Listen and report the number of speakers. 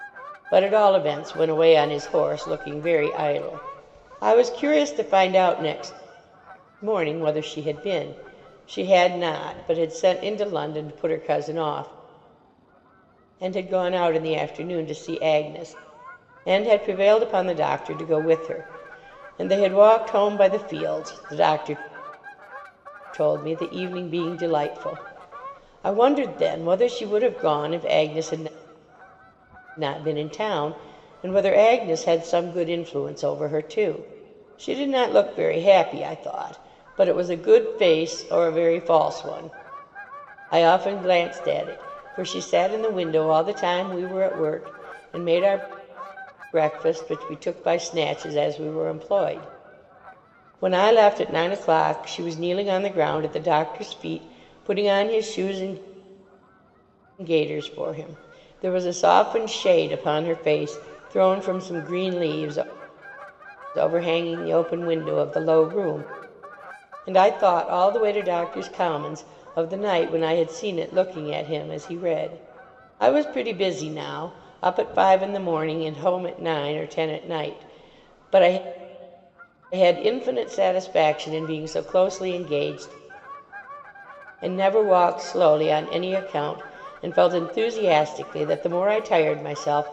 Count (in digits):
1